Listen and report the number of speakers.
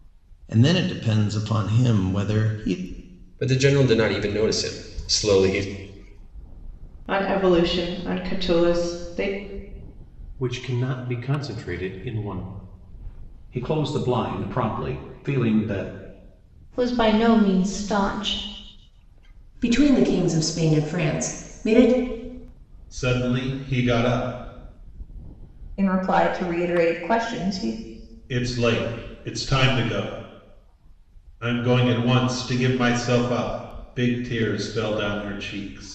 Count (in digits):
9